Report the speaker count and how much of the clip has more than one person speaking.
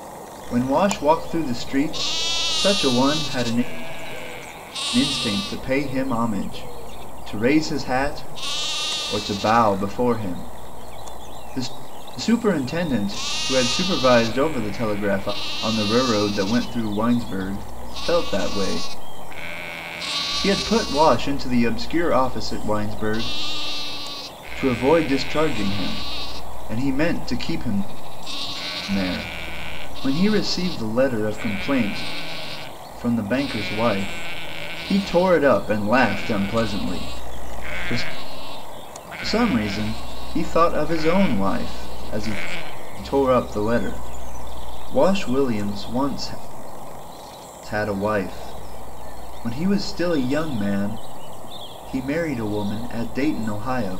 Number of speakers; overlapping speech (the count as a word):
one, no overlap